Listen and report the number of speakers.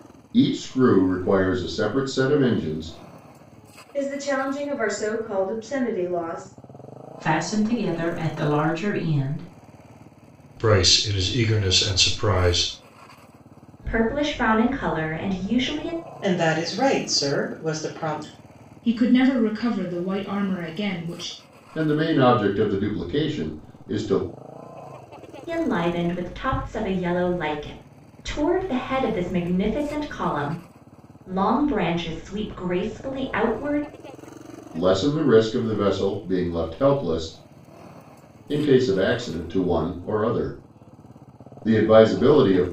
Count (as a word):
seven